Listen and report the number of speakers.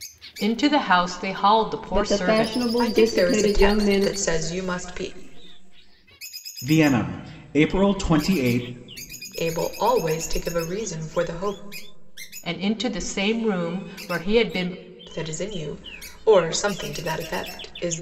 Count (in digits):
4